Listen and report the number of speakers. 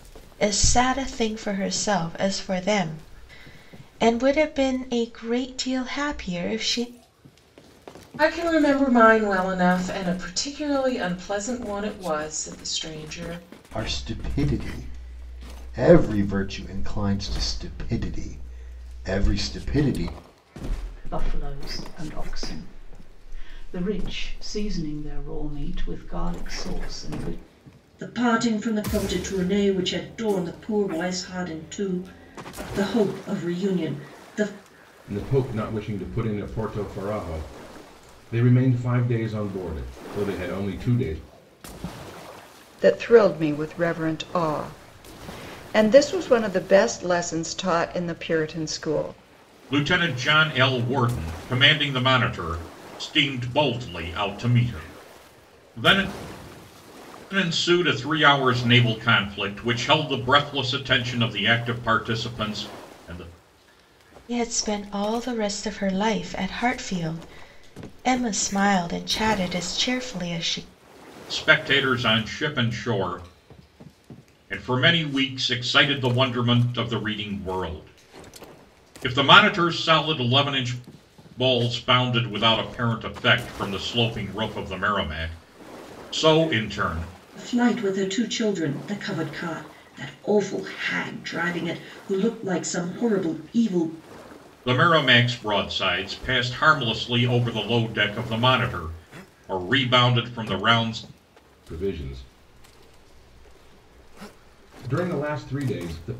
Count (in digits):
8